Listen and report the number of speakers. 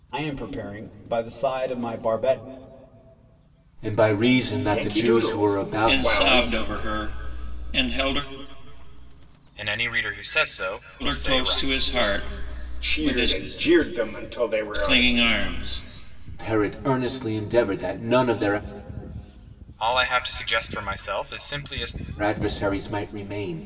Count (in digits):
5